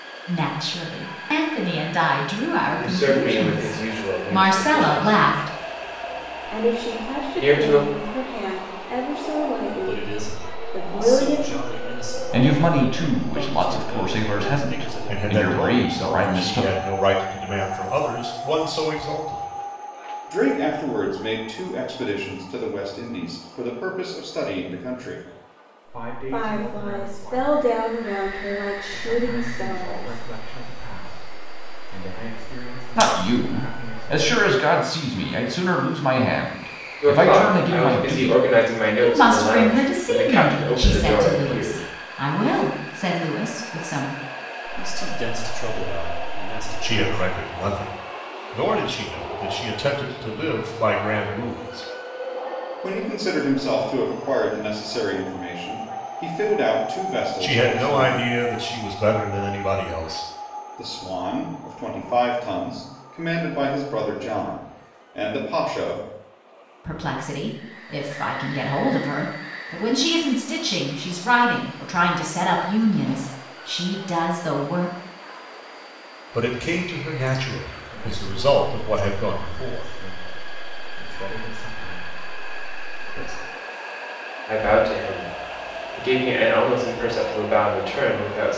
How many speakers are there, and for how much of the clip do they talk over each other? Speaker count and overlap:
8, about 25%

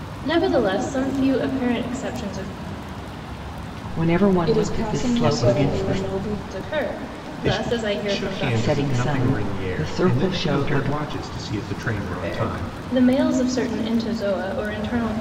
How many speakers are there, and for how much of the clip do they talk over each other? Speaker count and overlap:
4, about 44%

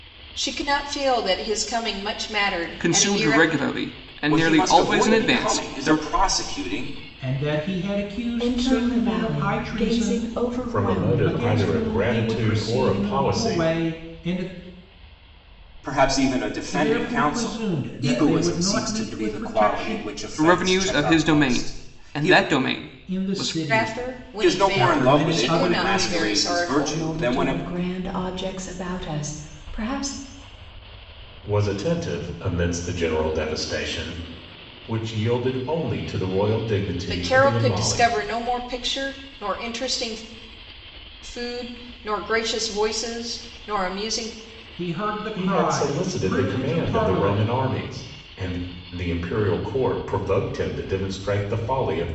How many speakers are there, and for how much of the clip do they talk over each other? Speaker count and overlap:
6, about 39%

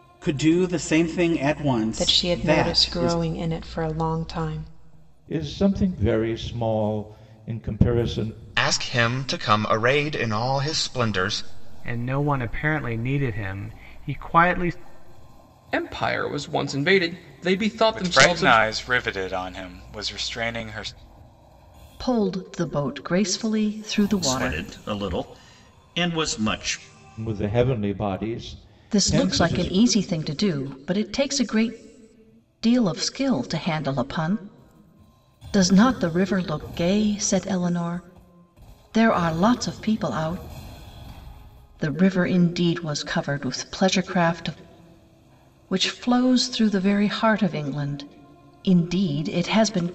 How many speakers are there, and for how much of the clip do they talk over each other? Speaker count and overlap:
9, about 7%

